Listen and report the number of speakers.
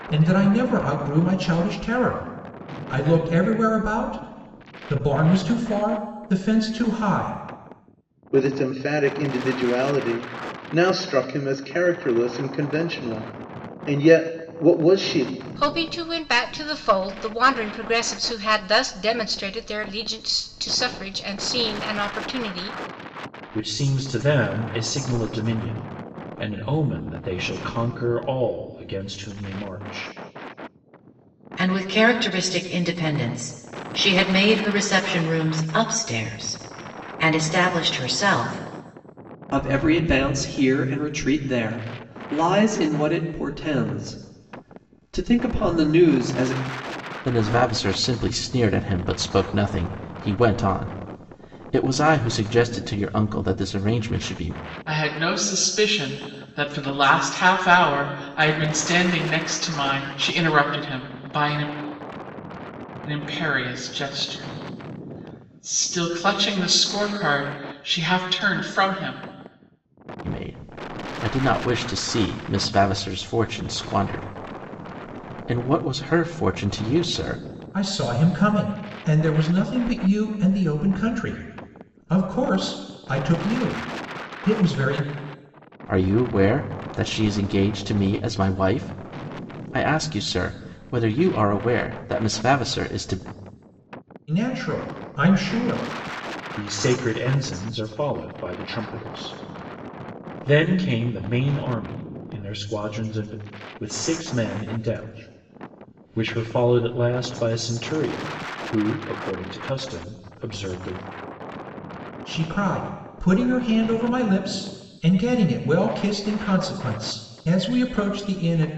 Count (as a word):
eight